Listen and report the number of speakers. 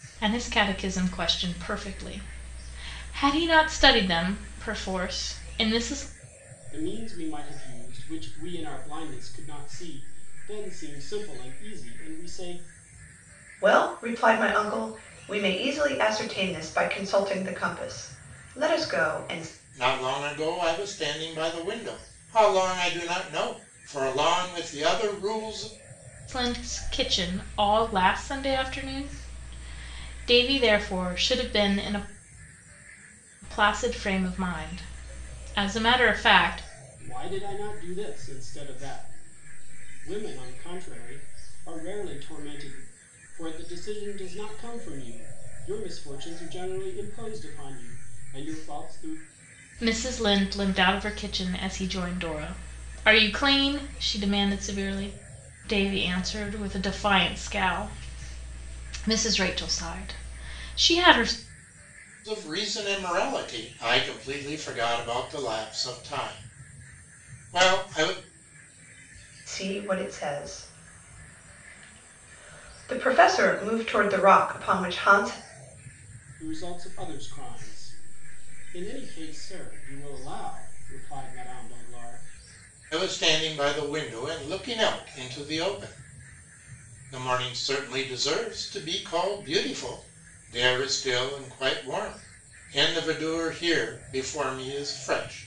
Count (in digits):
4